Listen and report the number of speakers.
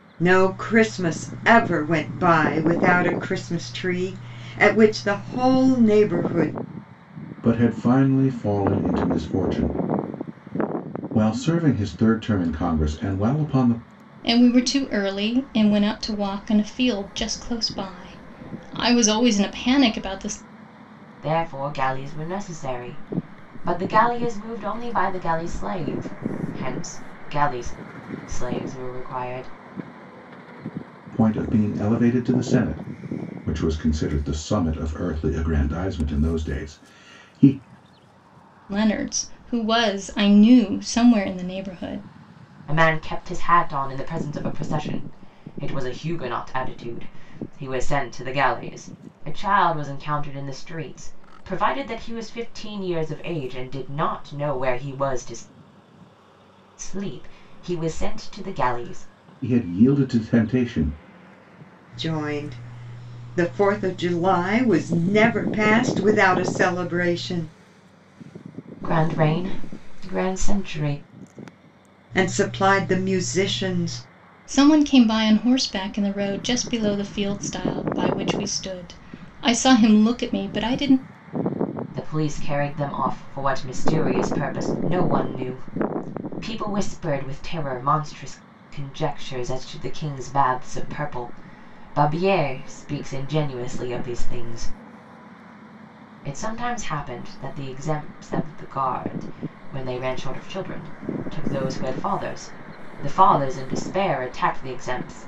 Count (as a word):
four